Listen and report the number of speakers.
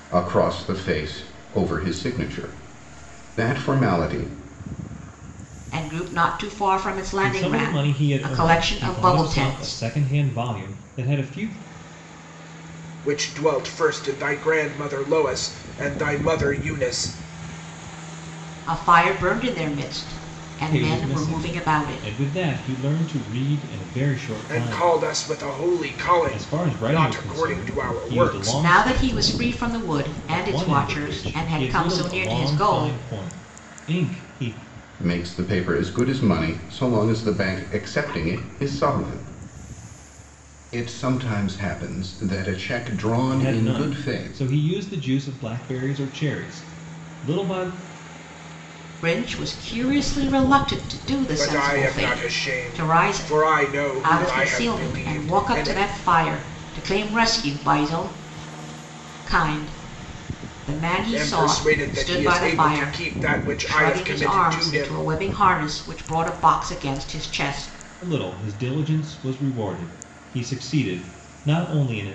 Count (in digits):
4